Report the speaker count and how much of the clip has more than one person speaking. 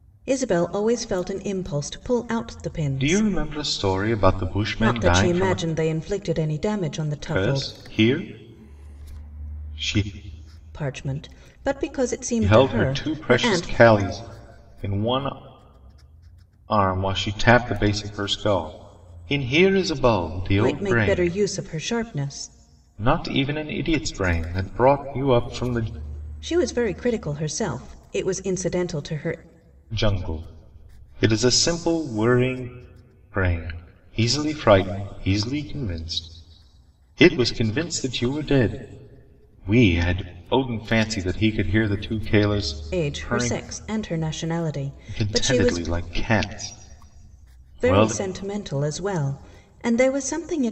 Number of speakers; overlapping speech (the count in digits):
2, about 11%